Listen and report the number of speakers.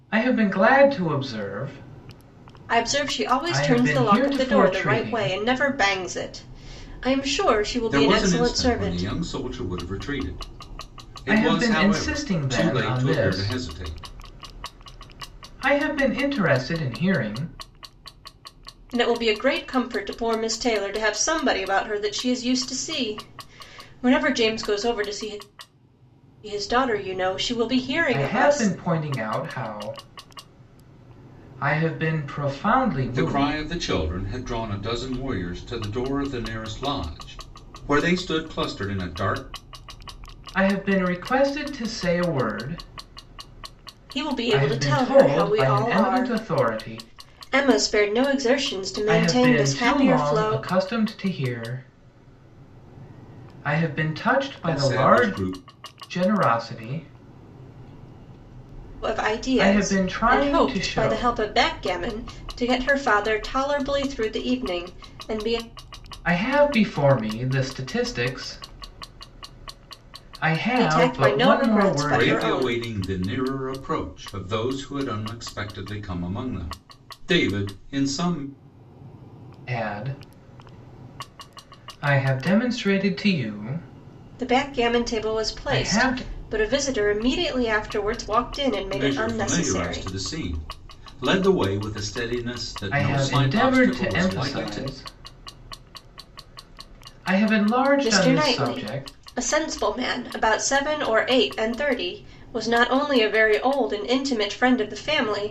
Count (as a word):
three